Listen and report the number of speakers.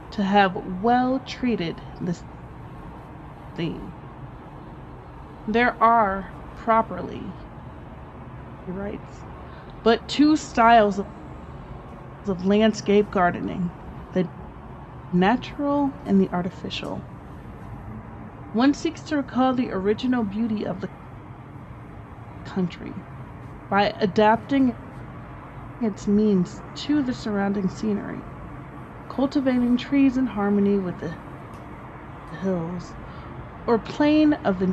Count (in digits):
1